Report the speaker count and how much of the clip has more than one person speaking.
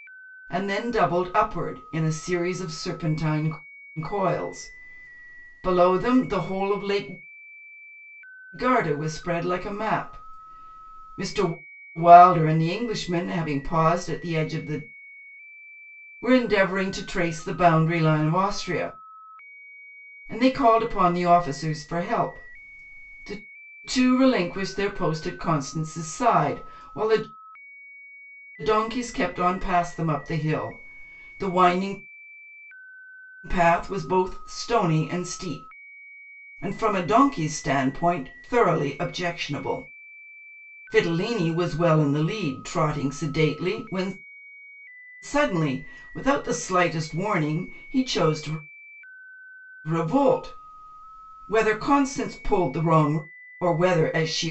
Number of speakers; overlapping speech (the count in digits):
1, no overlap